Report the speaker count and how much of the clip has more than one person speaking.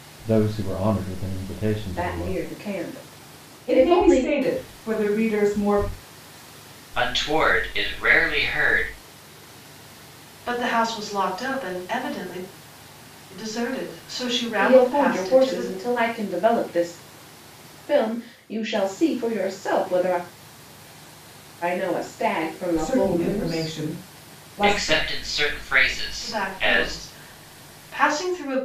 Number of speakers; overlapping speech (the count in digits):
5, about 15%